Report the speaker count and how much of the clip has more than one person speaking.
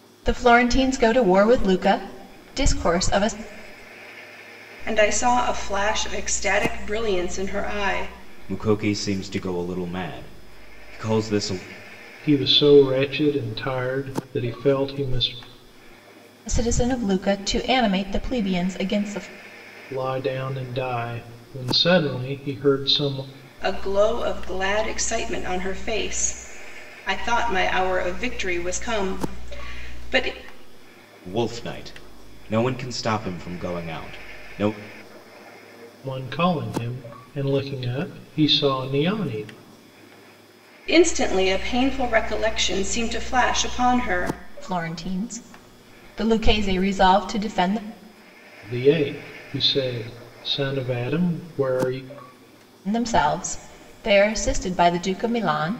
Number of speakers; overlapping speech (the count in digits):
4, no overlap